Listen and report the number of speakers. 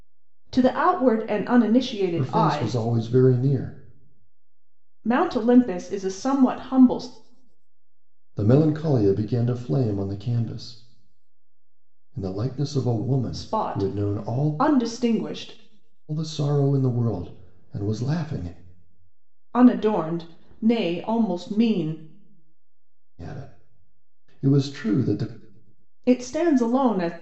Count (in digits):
2